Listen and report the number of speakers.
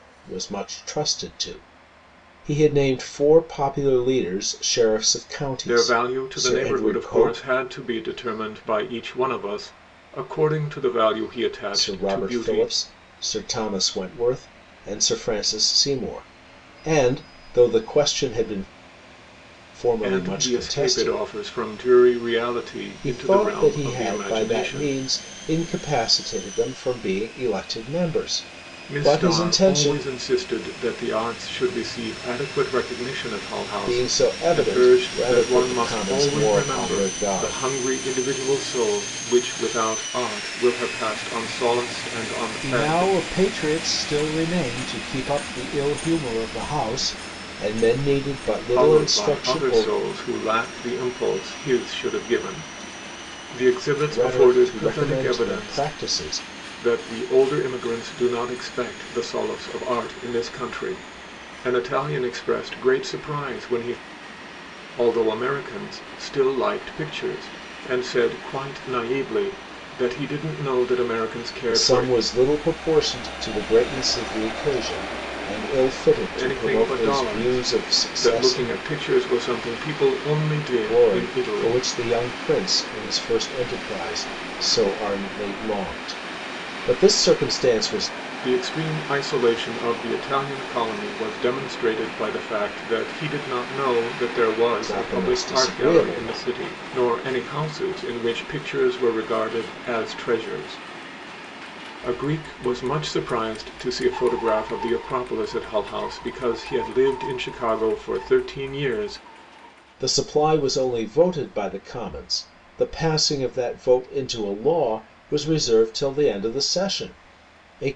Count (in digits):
2